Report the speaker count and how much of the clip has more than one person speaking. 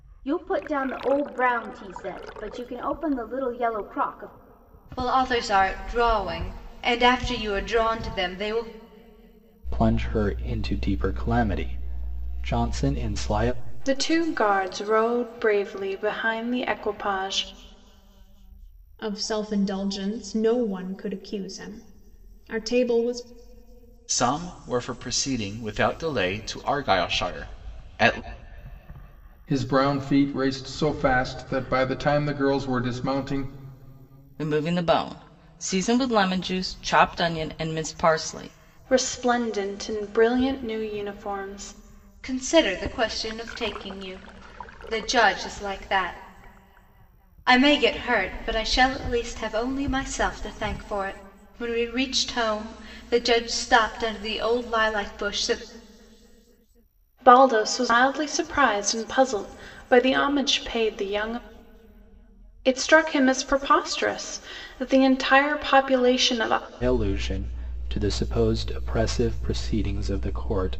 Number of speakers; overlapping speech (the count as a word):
eight, no overlap